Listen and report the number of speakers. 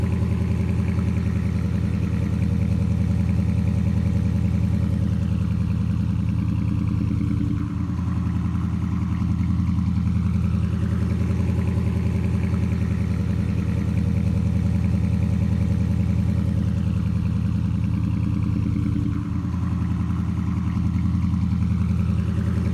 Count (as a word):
zero